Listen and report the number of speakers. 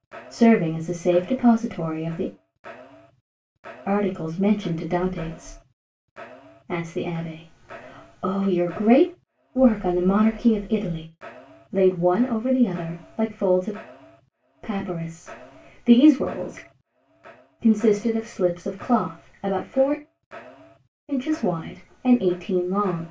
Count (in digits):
1